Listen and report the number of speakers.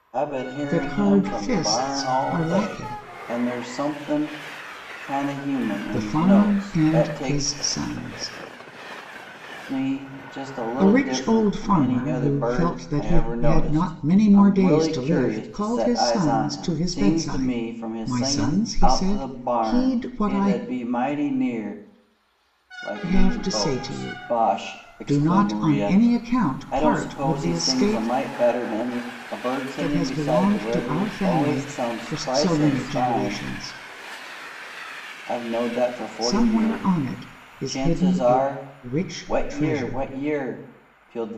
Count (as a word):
two